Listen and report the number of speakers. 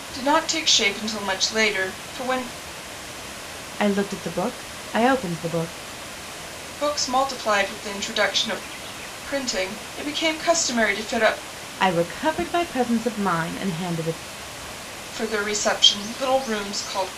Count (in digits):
2